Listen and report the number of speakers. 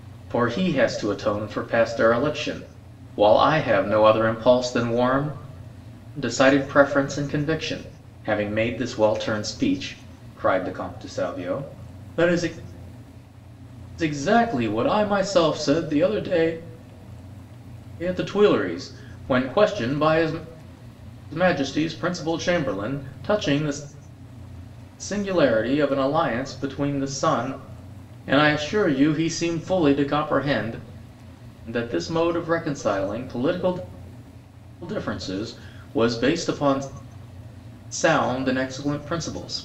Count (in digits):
1